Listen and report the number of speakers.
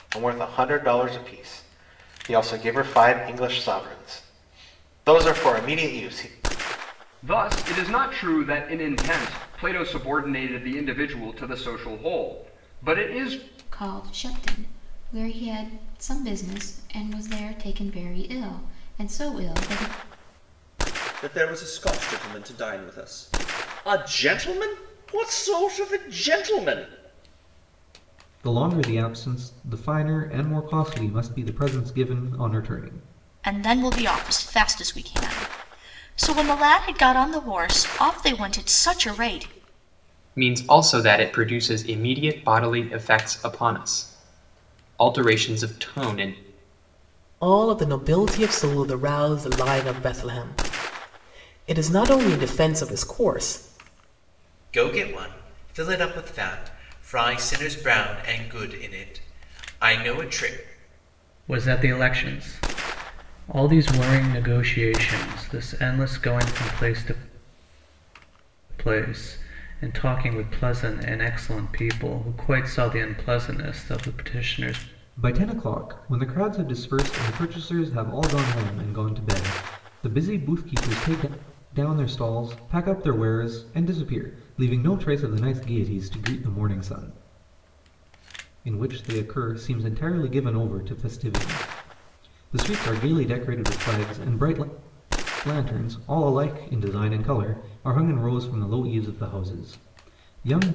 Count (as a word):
ten